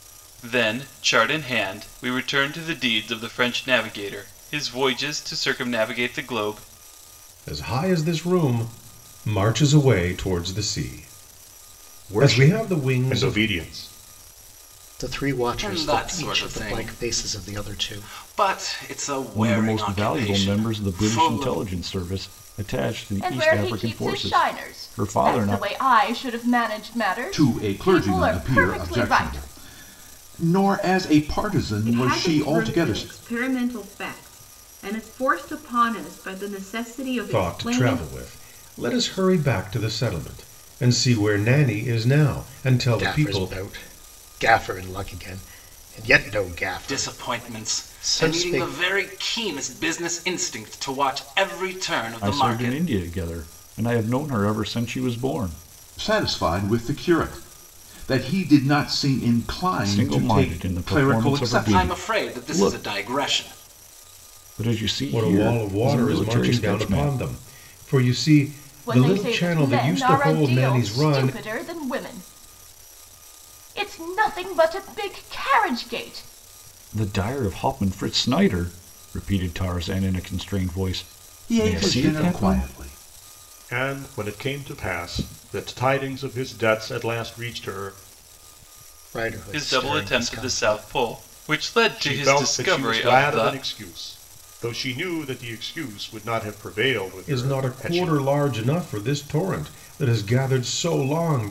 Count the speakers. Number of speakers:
nine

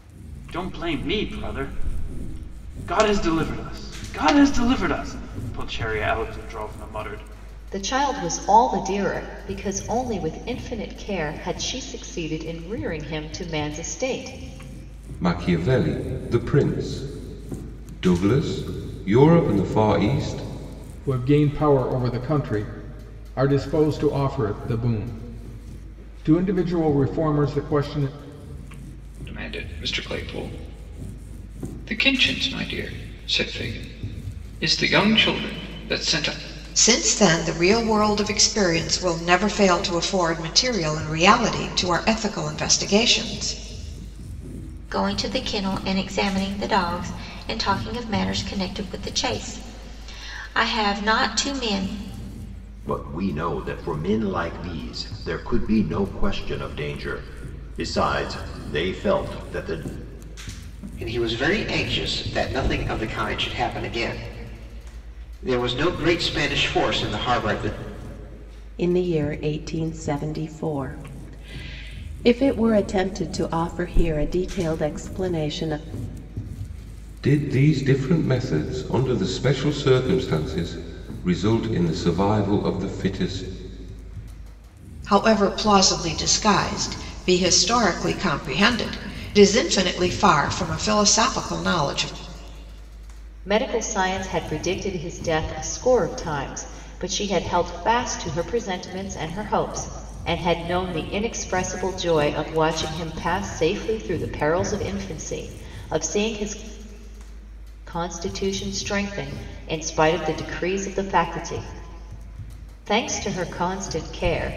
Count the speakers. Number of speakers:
ten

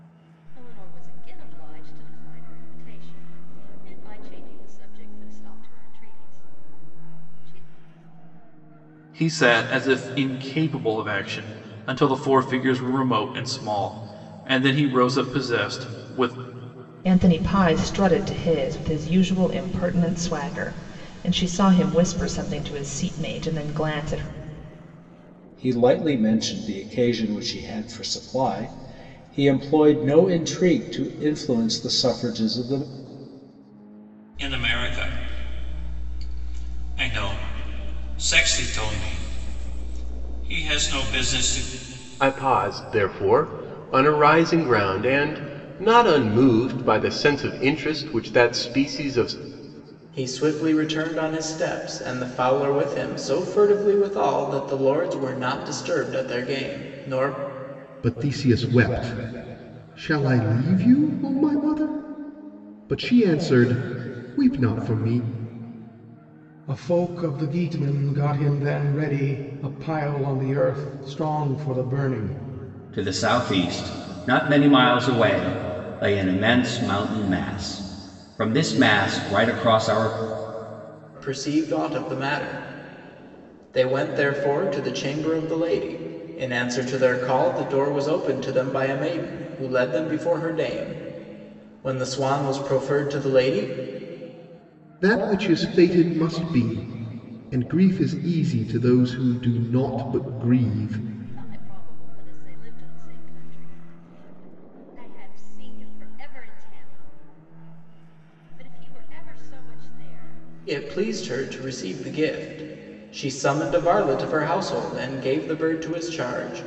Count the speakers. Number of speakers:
ten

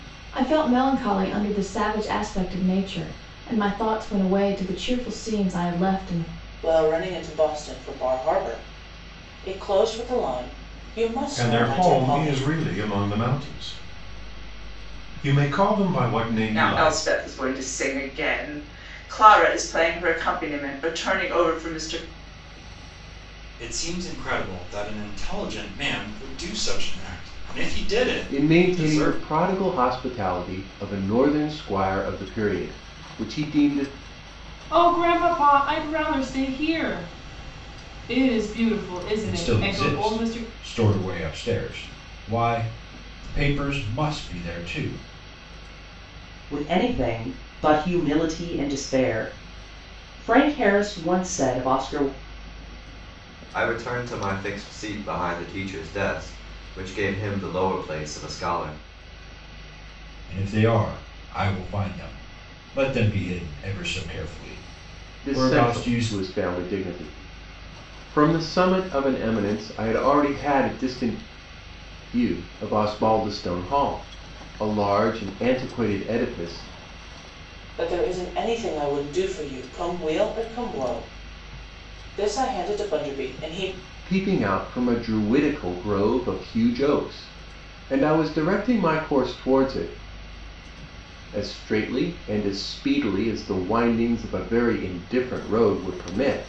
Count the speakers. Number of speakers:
ten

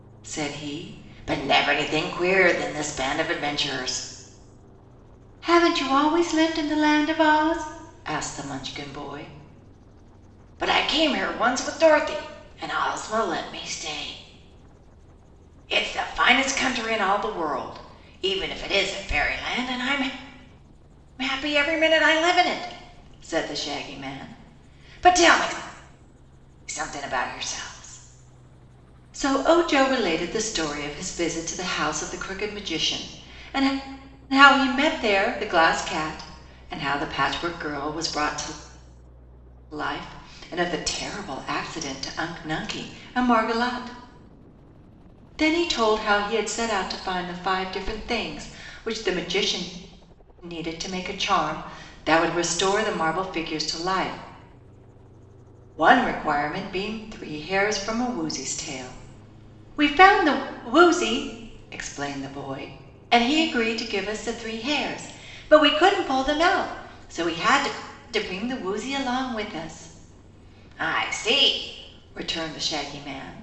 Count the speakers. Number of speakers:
one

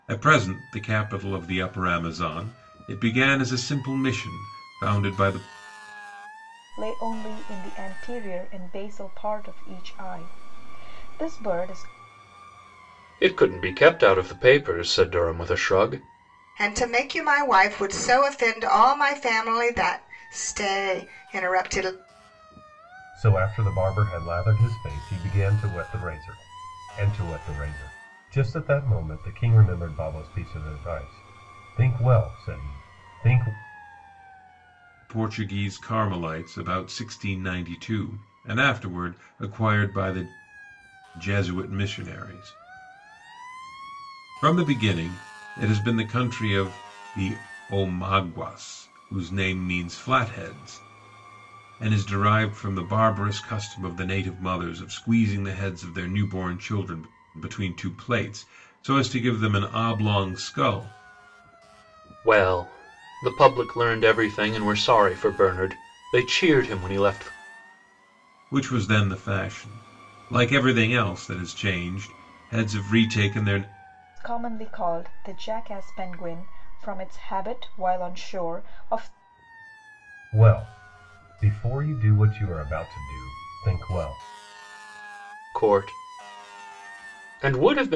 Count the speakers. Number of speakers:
five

